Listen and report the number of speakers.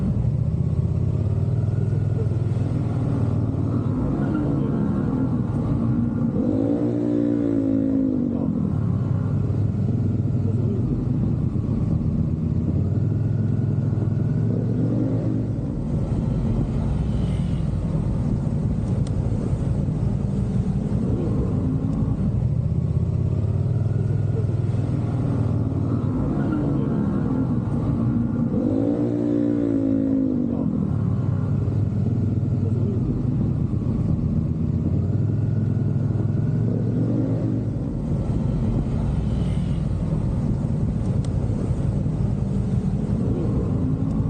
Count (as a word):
zero